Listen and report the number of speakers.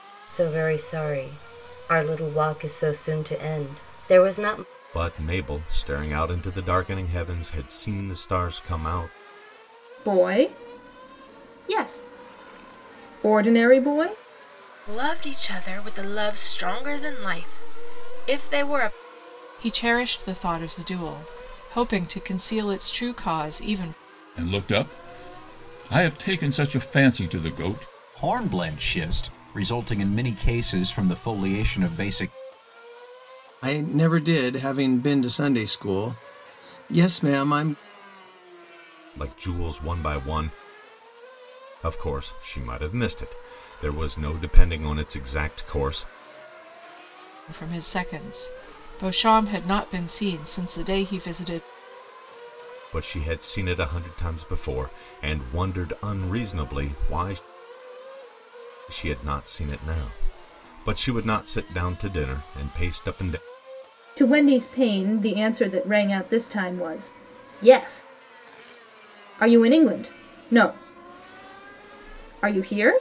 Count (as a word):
eight